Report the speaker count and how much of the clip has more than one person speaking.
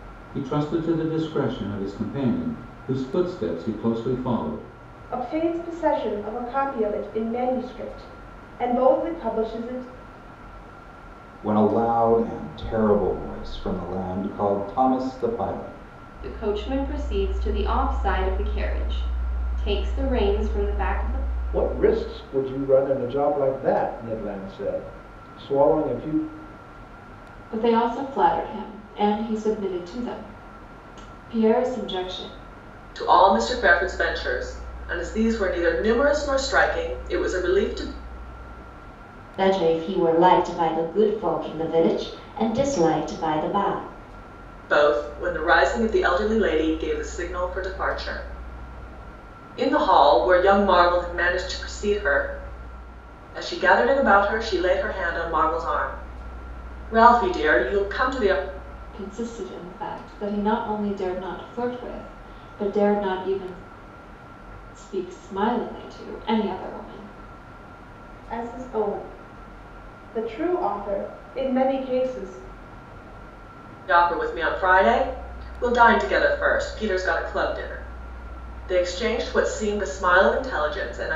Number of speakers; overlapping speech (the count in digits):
8, no overlap